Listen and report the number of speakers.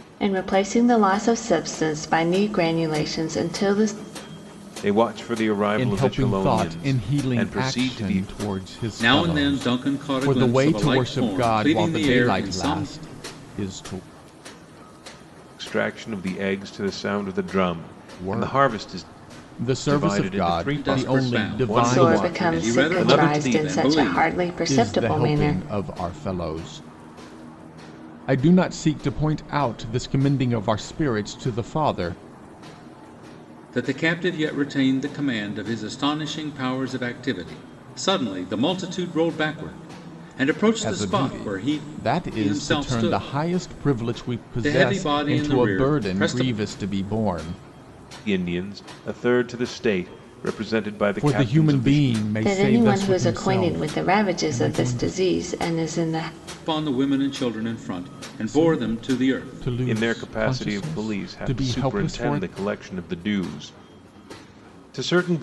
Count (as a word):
four